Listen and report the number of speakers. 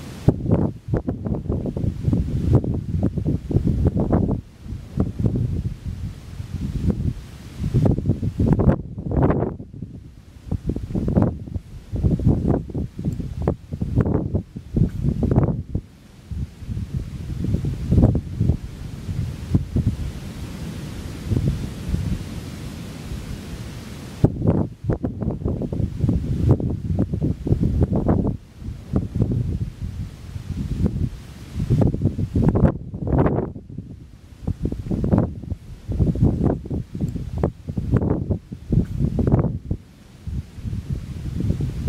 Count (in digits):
0